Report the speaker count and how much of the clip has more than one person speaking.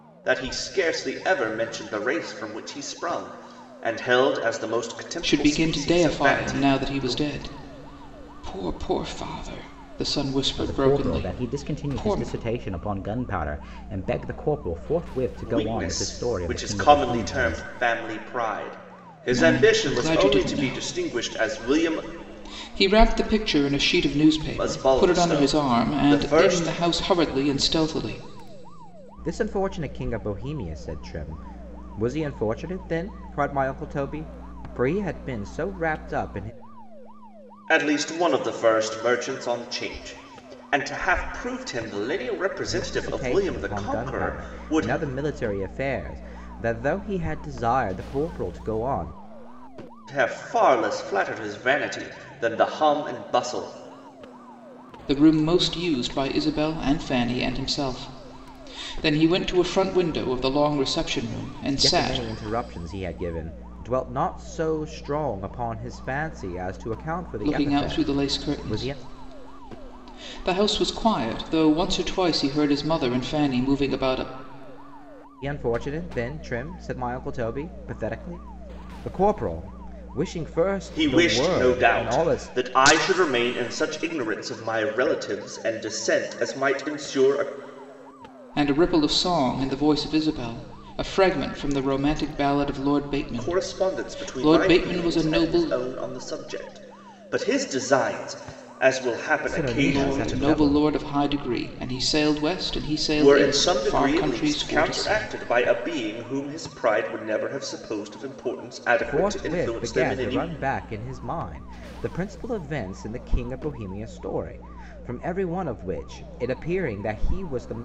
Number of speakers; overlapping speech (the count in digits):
3, about 21%